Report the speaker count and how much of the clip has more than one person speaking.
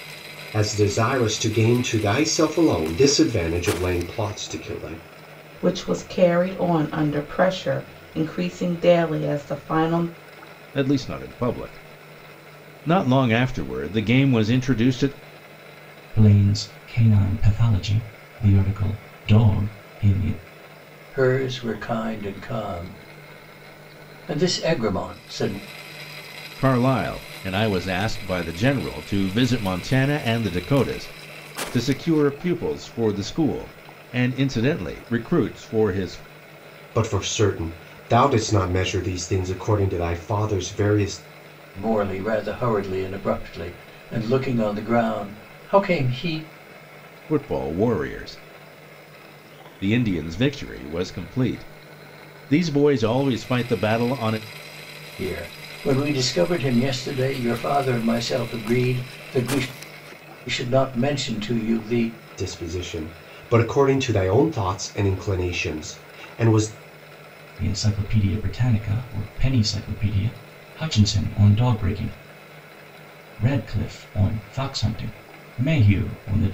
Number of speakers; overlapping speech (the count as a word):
five, no overlap